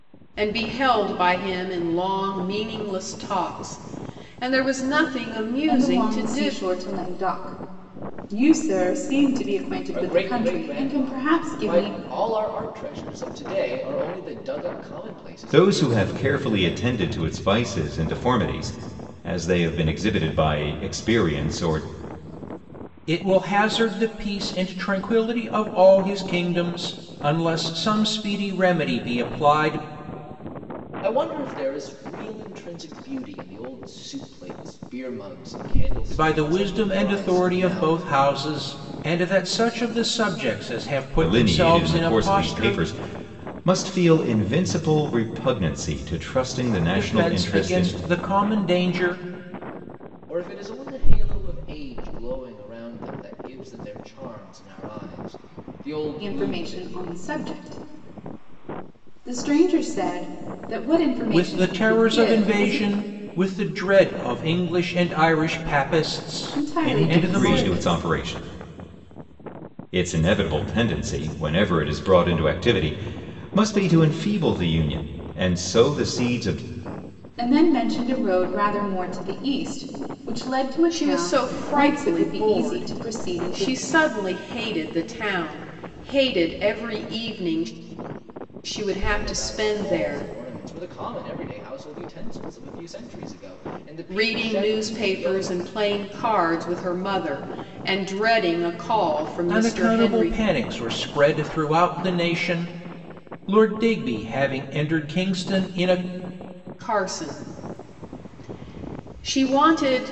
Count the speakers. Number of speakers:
5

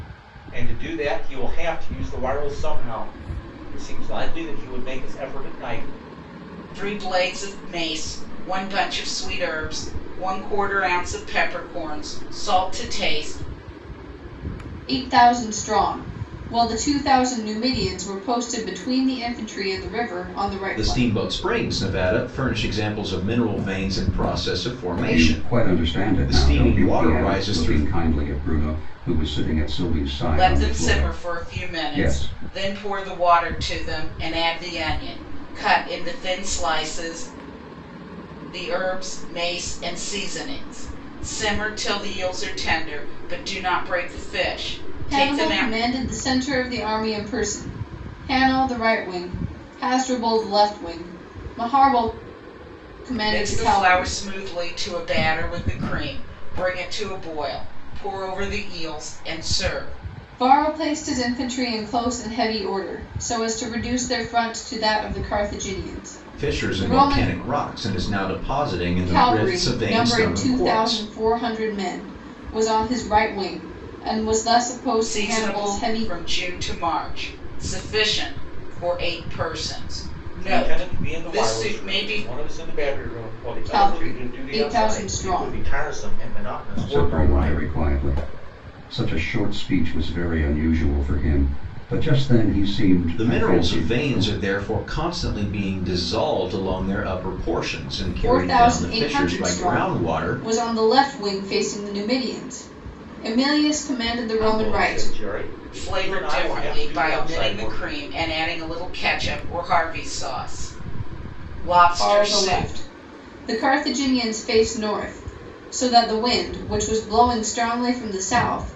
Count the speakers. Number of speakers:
5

